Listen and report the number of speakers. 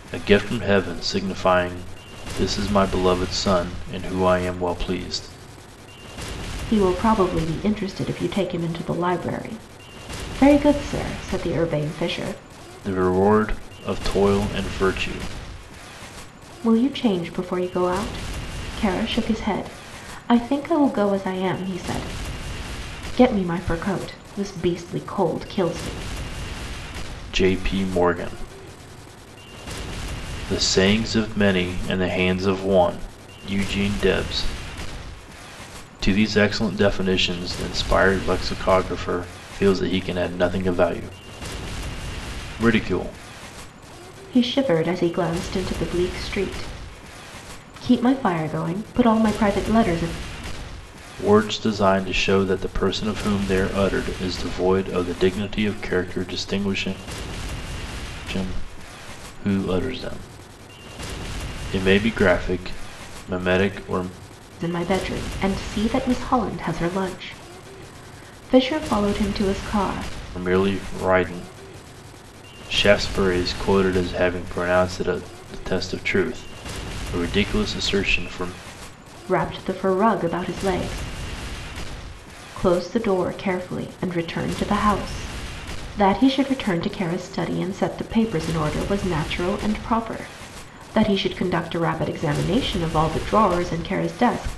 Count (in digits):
2